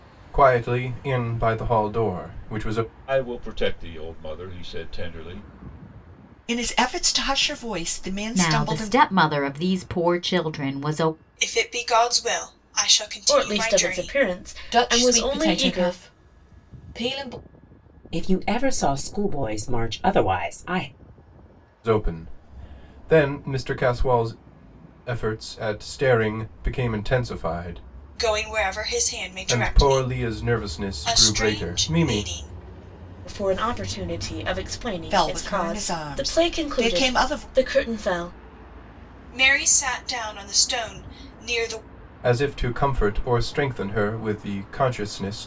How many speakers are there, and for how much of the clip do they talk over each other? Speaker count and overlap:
8, about 16%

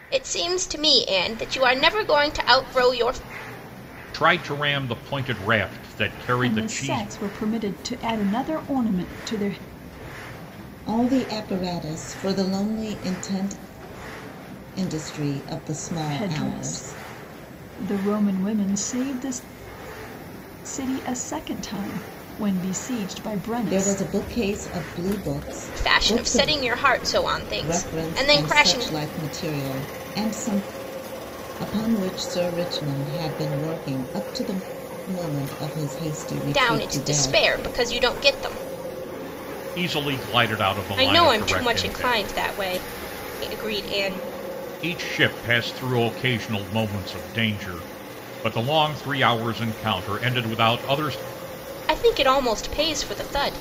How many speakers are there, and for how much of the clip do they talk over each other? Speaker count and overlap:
4, about 12%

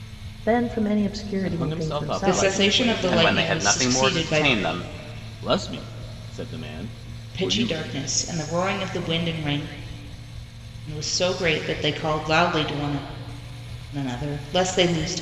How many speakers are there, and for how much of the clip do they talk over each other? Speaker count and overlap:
4, about 24%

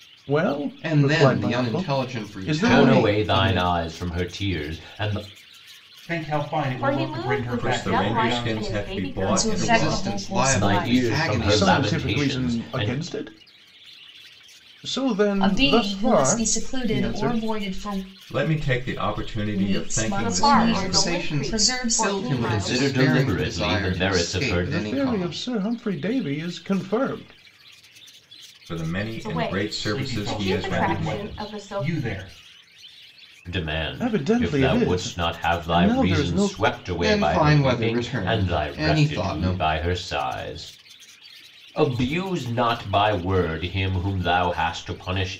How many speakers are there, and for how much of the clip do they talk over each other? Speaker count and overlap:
7, about 55%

